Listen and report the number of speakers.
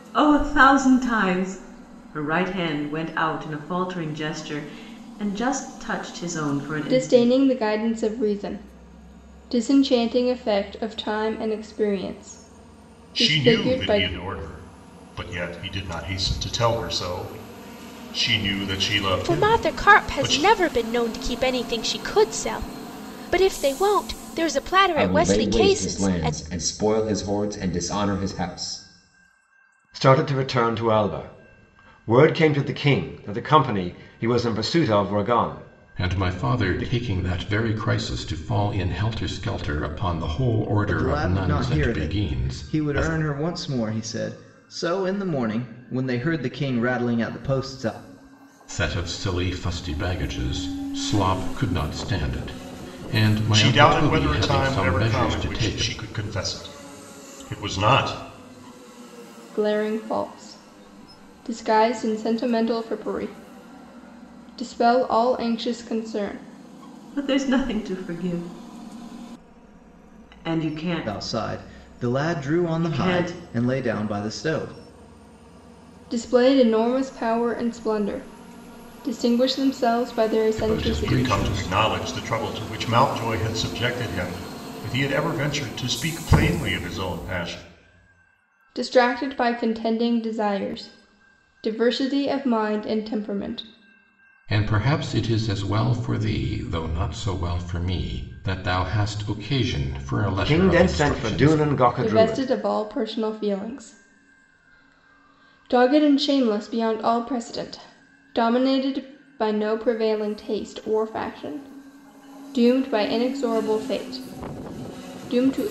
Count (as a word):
eight